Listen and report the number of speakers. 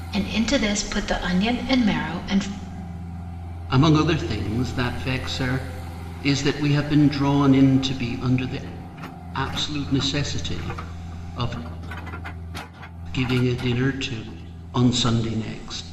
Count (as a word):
two